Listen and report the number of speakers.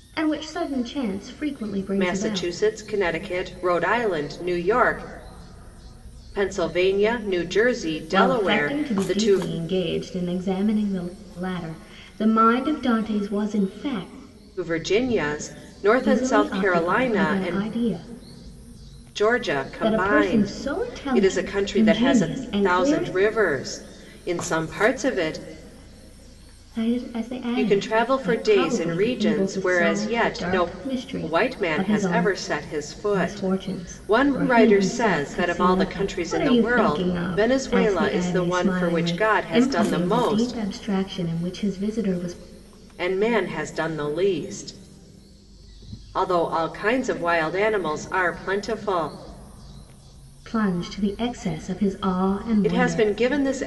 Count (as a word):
two